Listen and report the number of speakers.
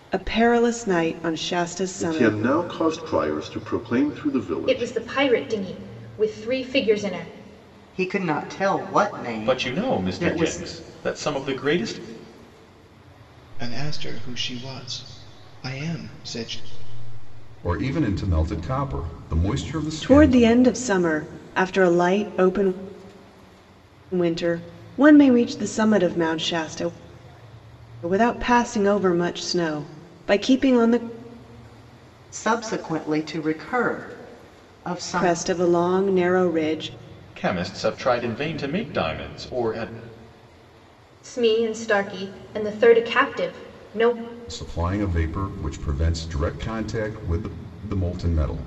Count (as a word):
seven